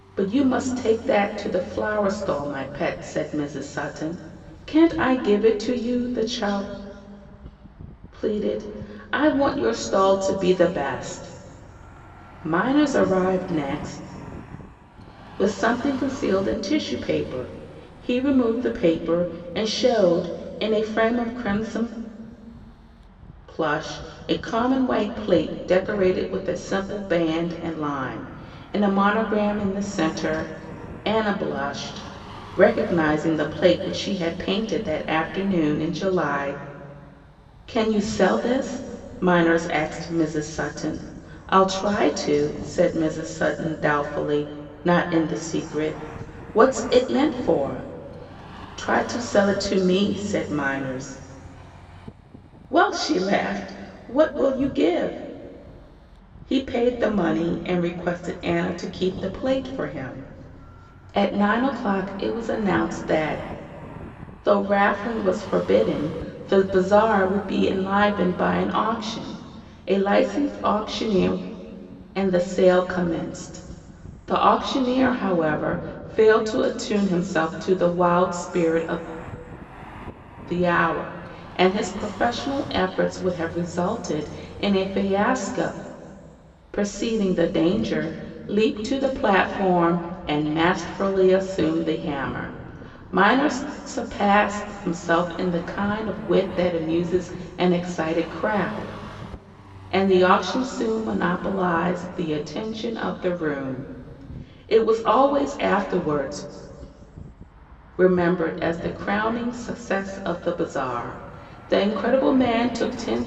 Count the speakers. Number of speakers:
1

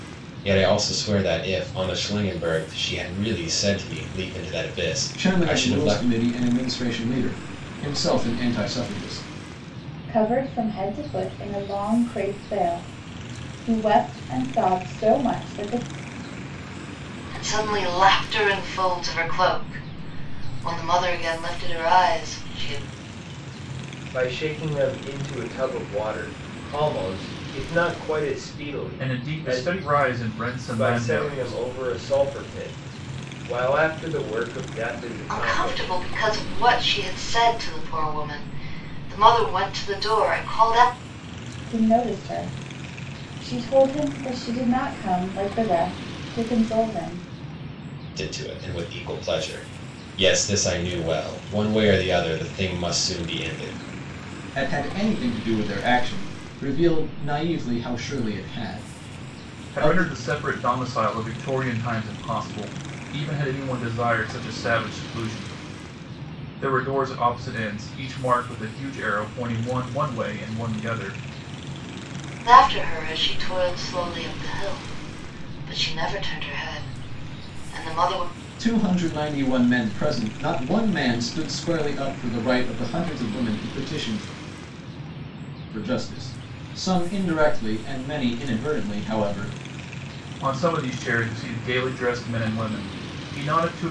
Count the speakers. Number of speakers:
6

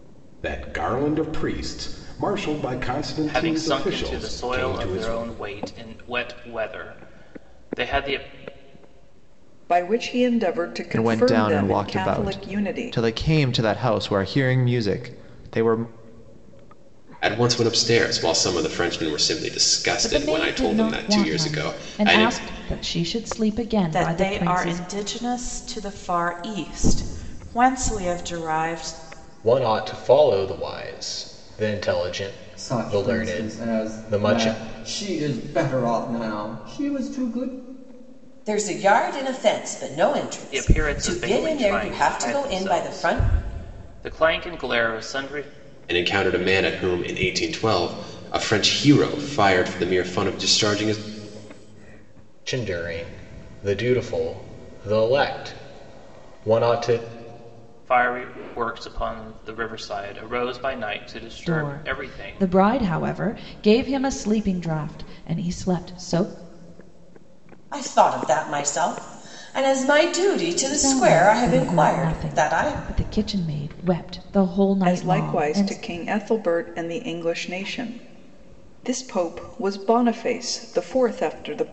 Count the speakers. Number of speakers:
10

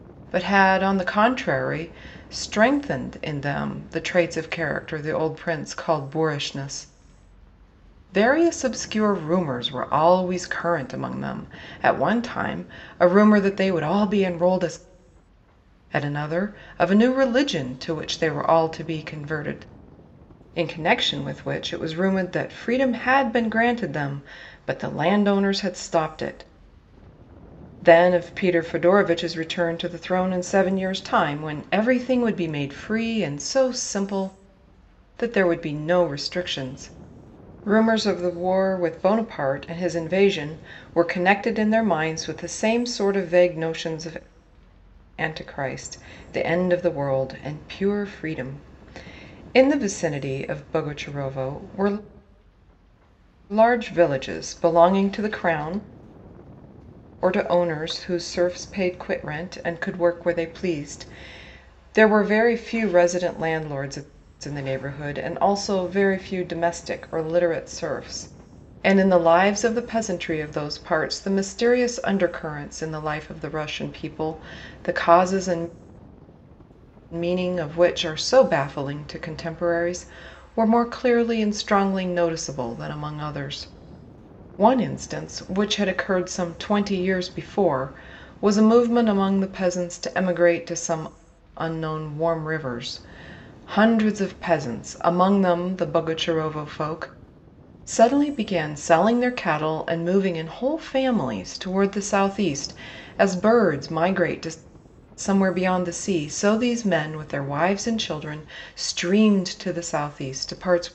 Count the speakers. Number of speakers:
1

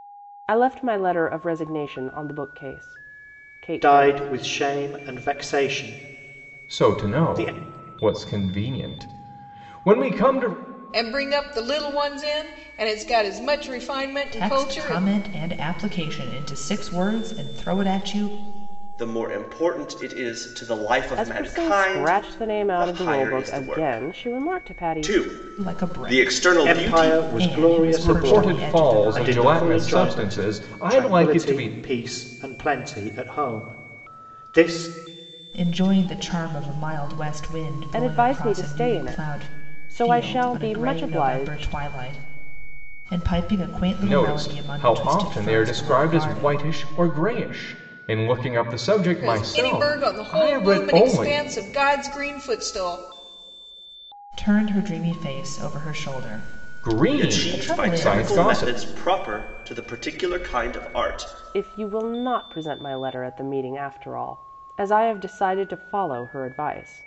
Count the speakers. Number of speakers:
6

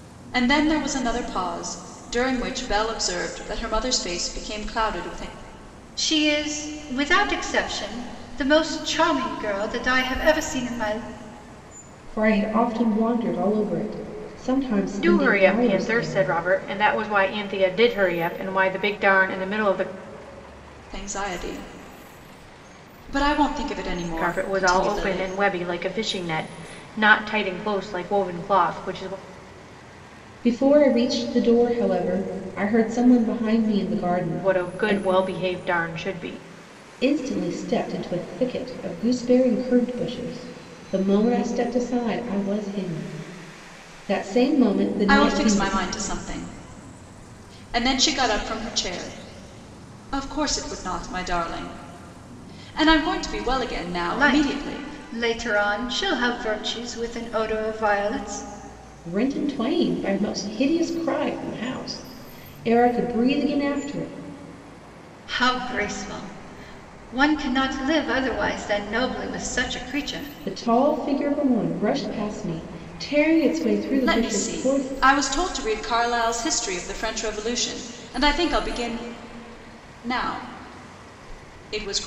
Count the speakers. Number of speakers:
4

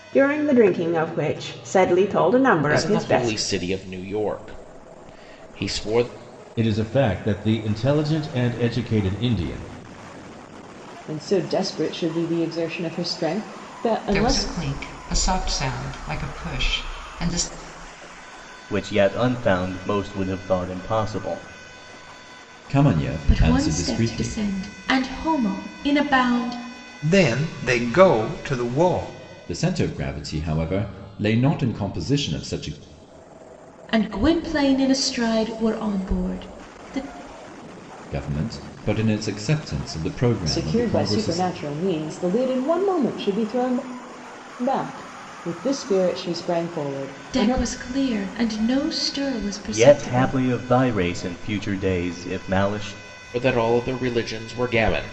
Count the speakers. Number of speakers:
9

